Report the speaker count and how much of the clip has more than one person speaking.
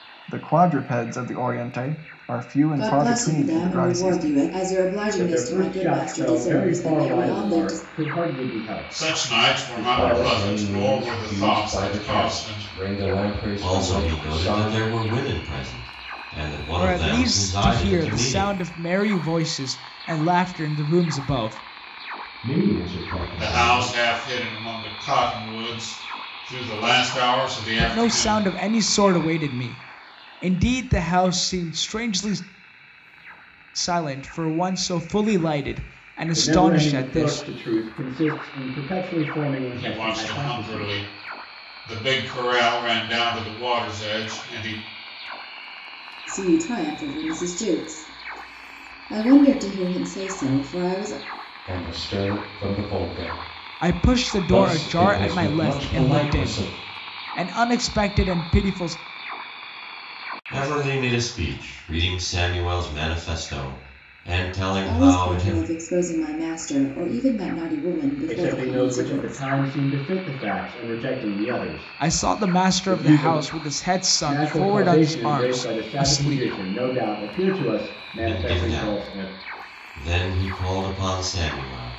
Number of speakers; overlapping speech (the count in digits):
8, about 31%